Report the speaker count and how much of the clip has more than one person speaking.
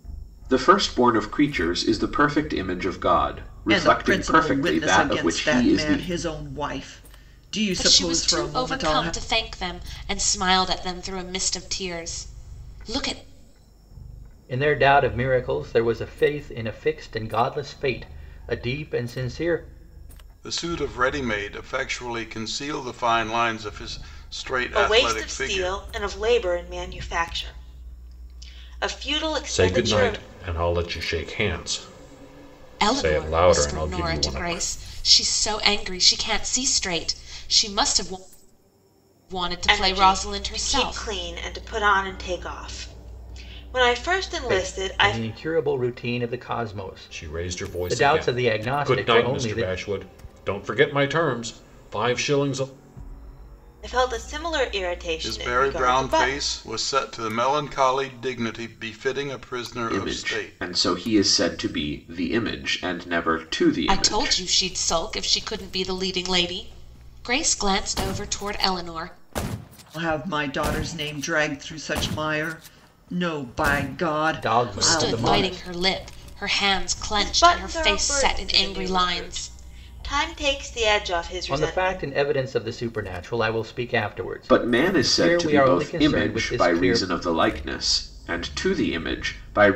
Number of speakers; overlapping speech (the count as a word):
seven, about 25%